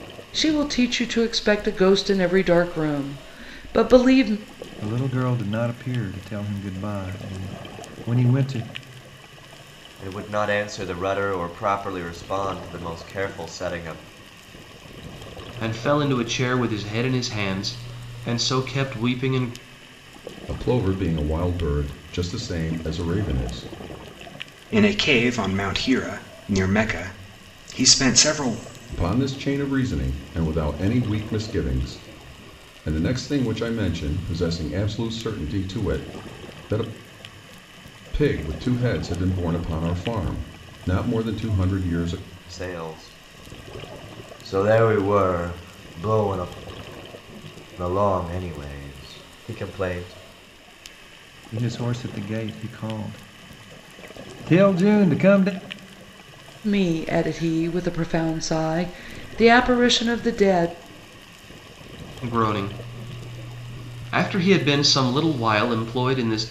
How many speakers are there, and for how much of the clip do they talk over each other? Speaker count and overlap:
6, no overlap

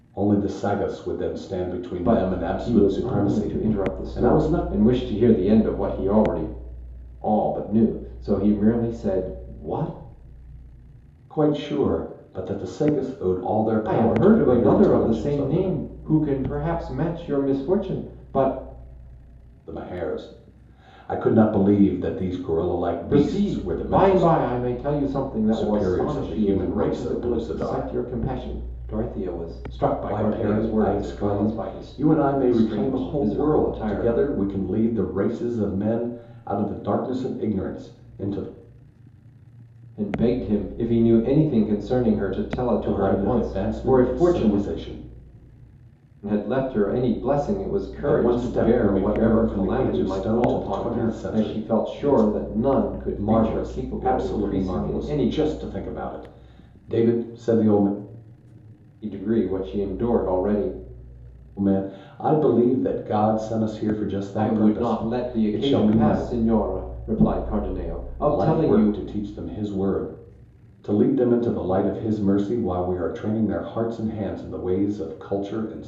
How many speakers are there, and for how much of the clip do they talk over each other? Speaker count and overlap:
2, about 30%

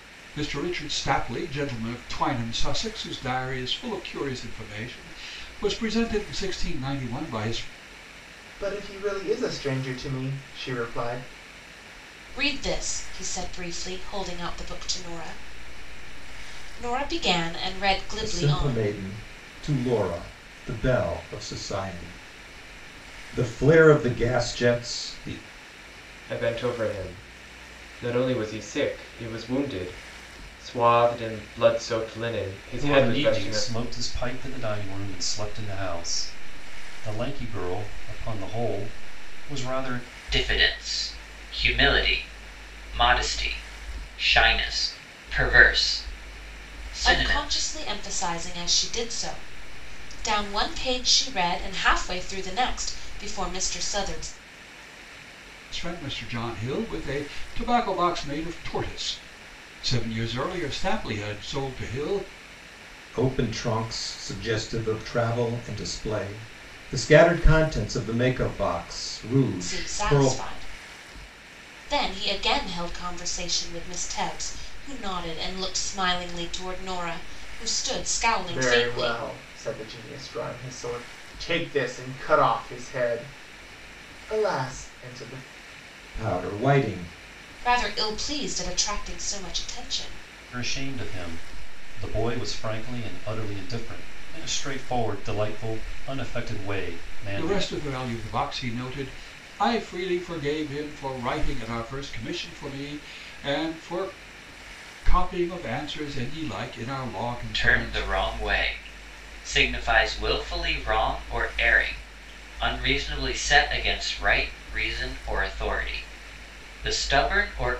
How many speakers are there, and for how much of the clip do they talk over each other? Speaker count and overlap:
7, about 4%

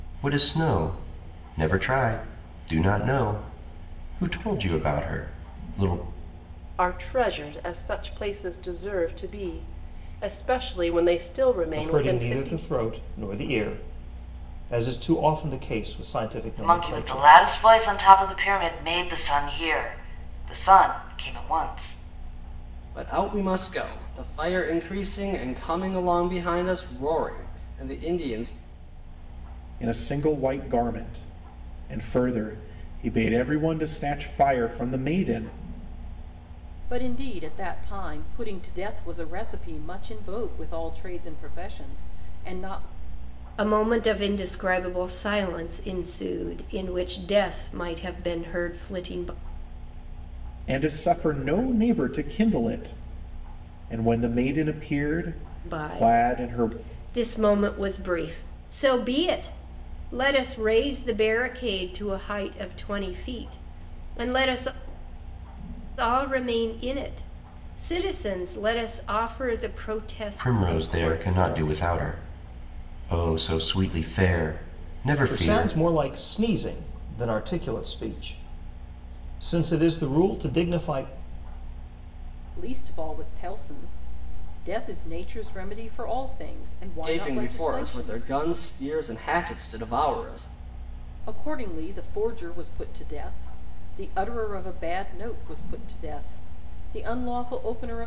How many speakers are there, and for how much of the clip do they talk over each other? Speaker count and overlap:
8, about 6%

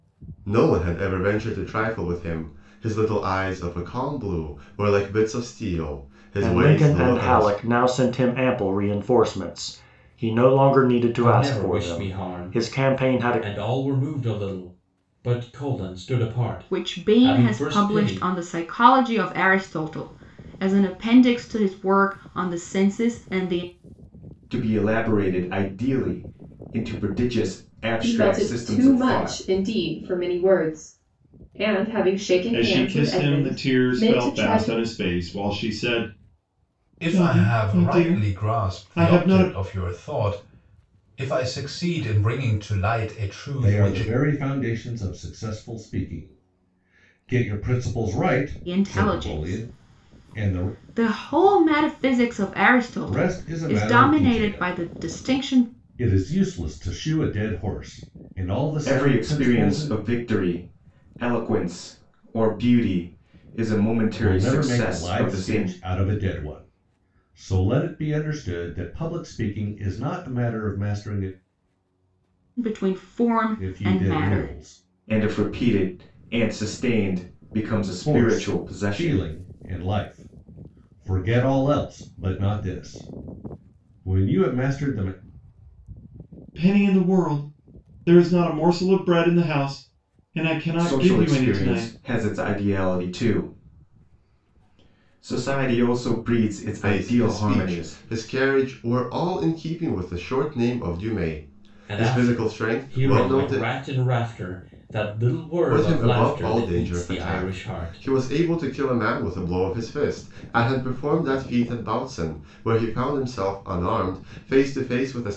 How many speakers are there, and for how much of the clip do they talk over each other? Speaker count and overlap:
9, about 25%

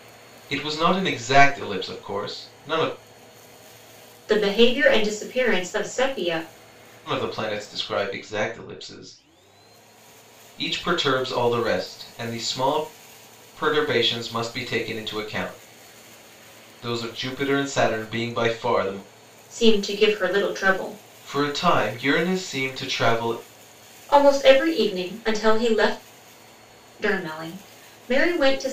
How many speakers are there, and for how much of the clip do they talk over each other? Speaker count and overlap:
2, no overlap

